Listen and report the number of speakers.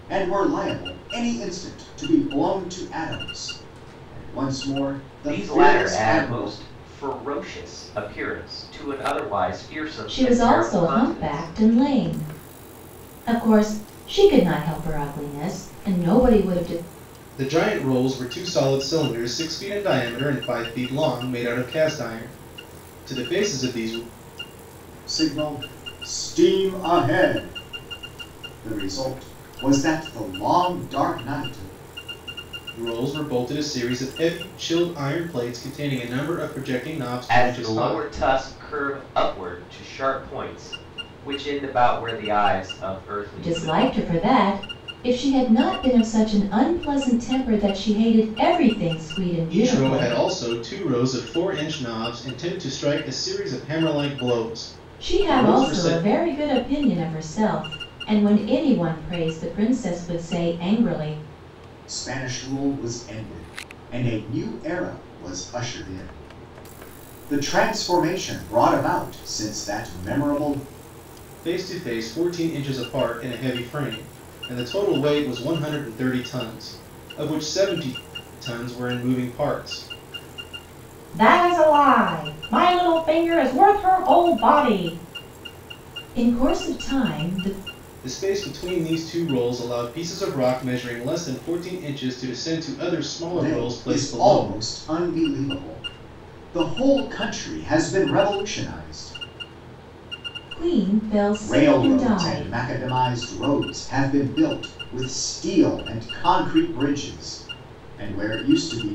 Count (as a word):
four